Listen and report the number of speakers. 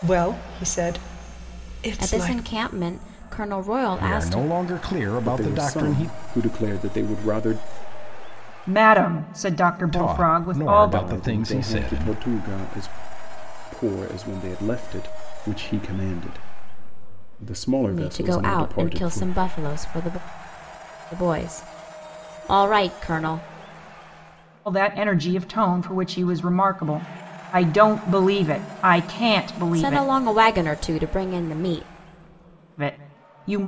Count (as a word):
five